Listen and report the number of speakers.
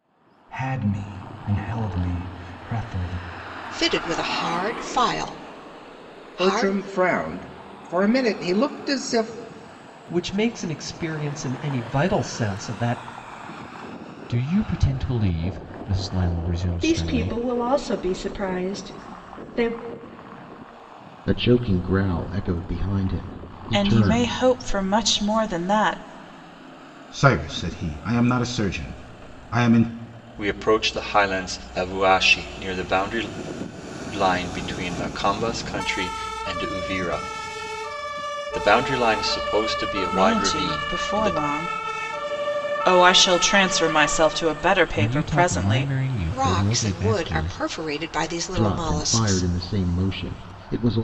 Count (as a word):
ten